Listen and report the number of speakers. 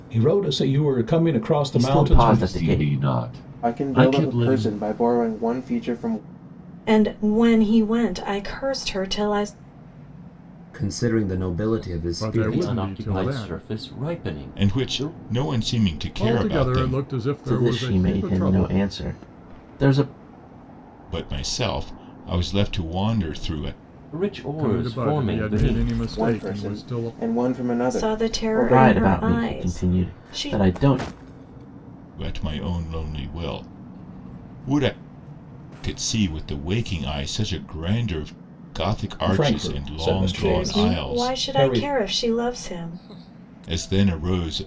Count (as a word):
nine